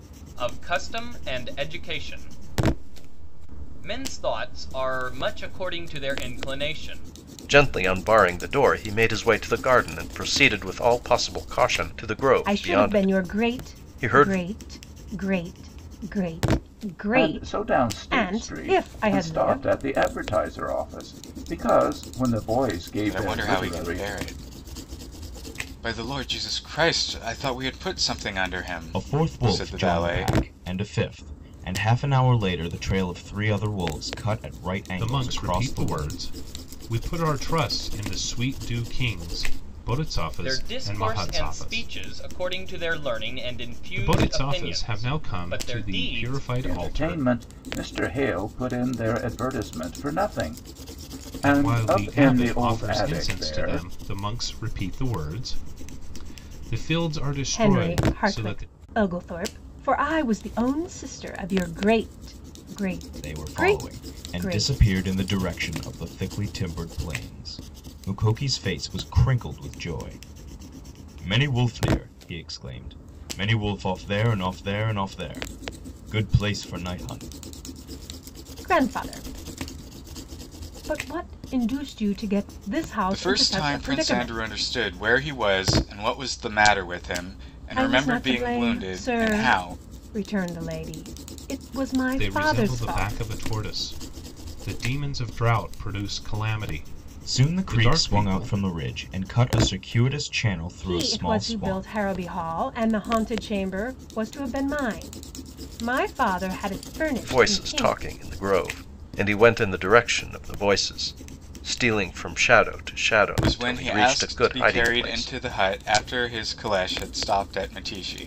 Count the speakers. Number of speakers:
7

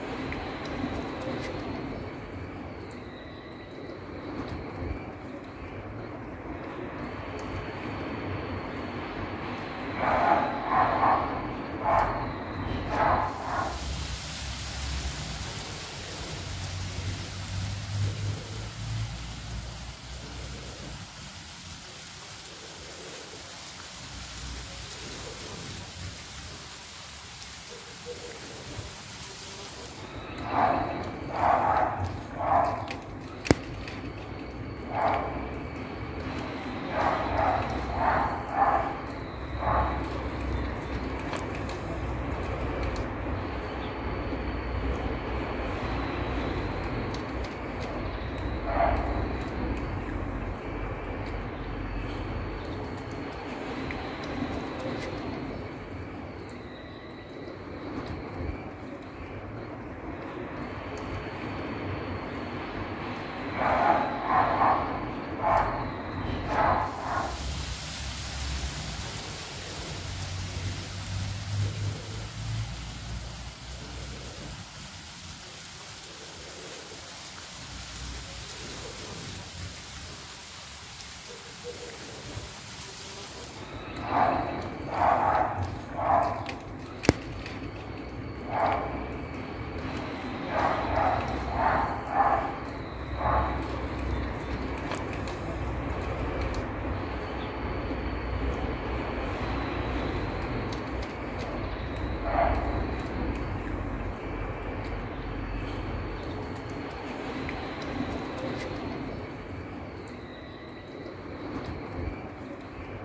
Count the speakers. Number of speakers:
0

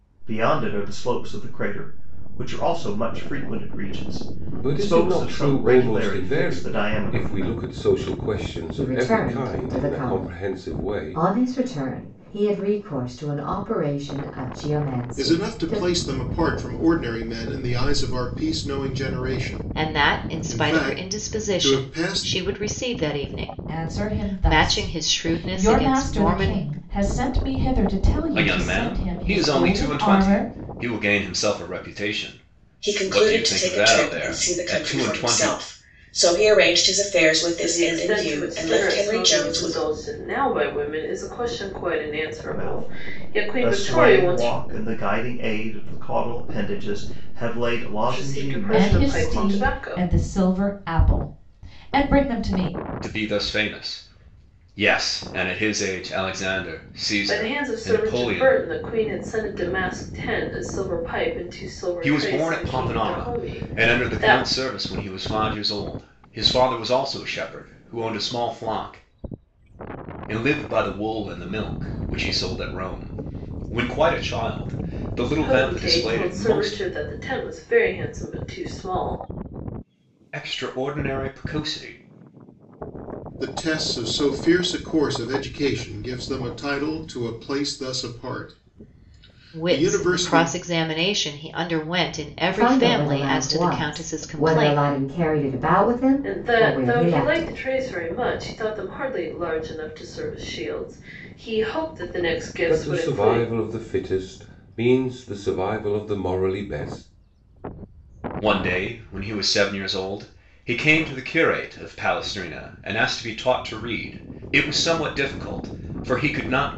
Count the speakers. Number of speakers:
9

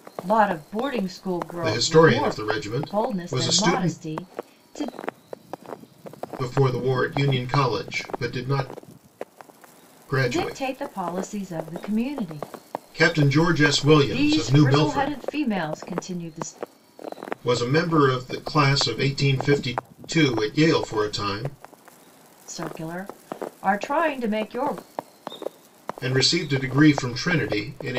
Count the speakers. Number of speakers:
2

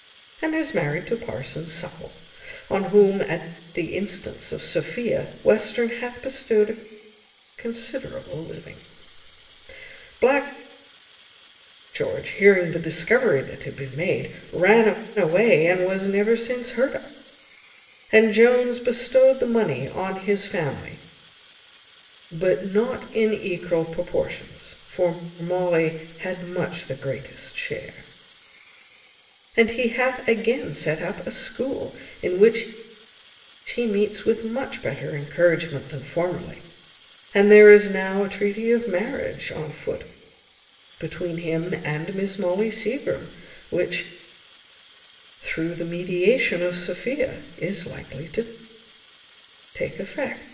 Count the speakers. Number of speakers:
1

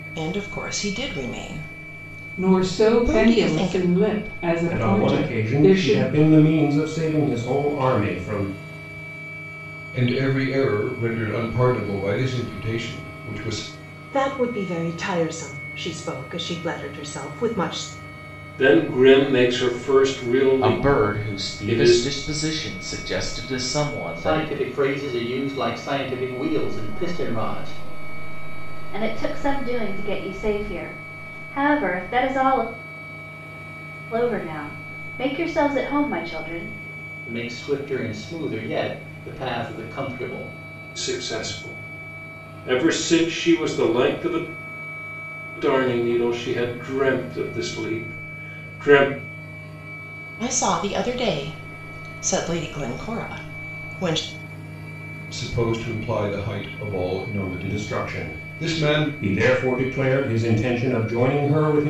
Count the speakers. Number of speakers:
10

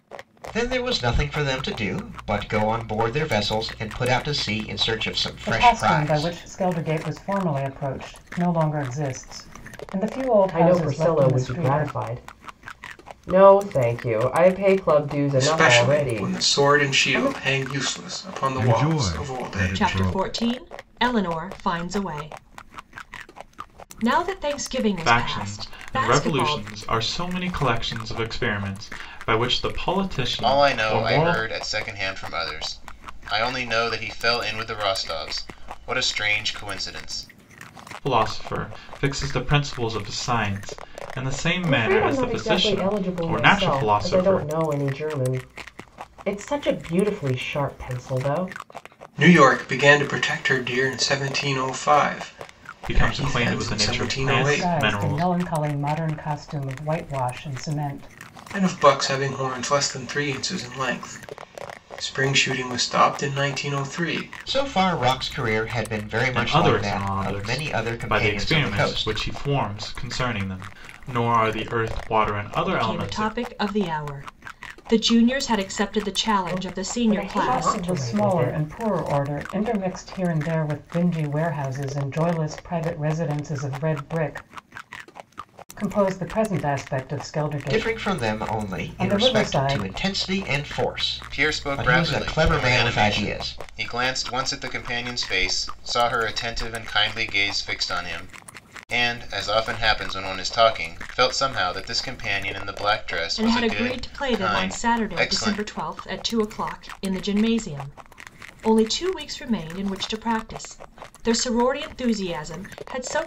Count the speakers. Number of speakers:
8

